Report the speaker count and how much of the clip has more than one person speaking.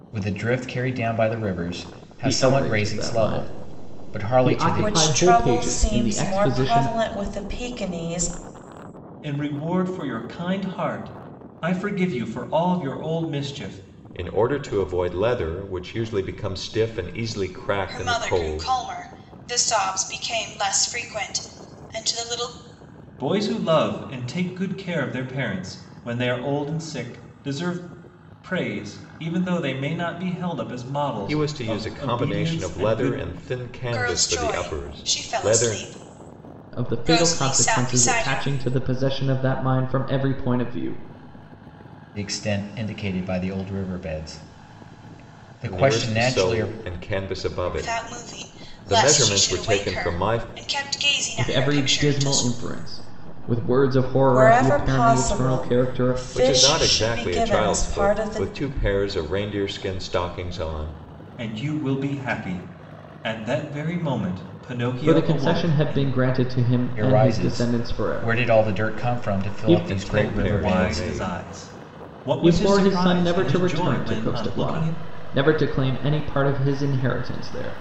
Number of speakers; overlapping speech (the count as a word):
six, about 37%